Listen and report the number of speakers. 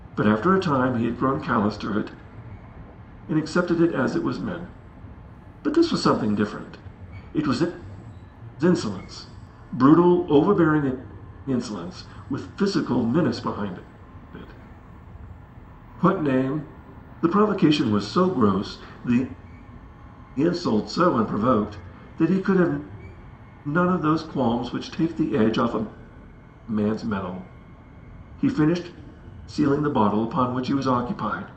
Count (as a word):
one